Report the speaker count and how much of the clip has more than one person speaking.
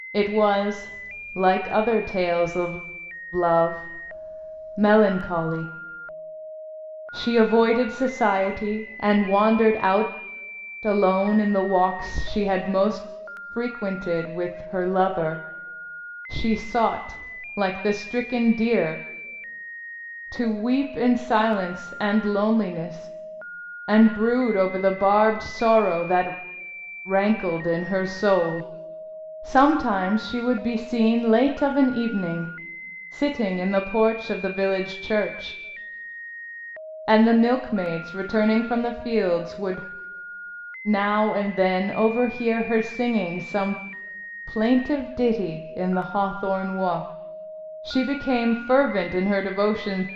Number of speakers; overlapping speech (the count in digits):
1, no overlap